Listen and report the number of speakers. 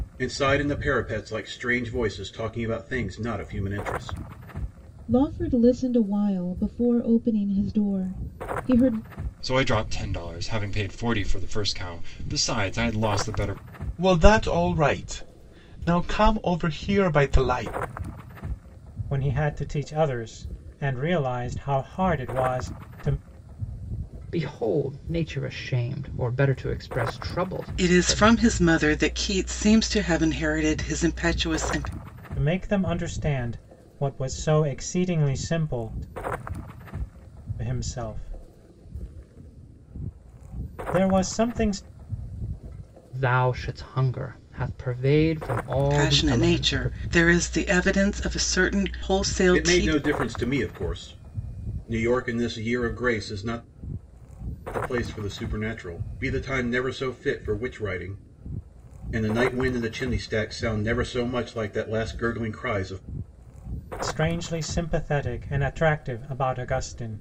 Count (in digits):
7